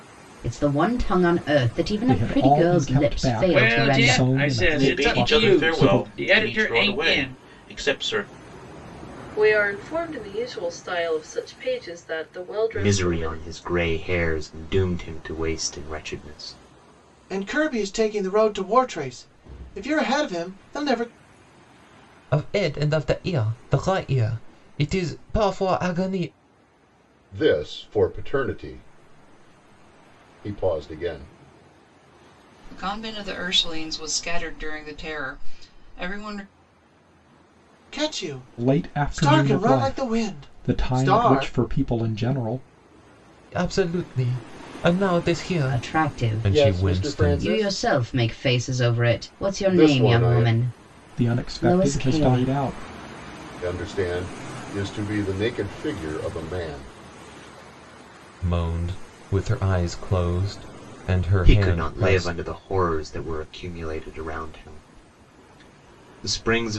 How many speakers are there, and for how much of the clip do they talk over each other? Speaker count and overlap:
10, about 24%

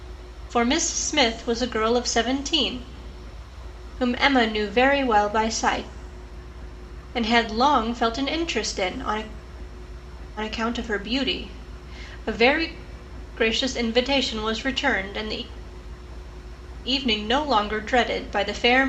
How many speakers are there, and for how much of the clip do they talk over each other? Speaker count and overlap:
1, no overlap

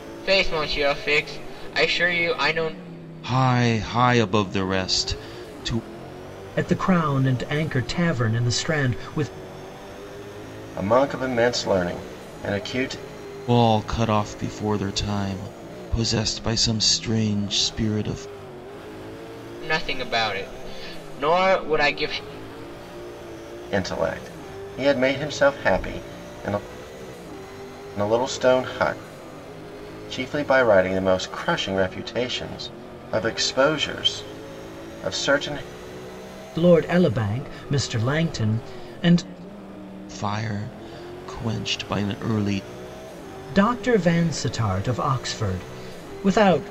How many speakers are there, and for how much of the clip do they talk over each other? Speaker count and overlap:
4, no overlap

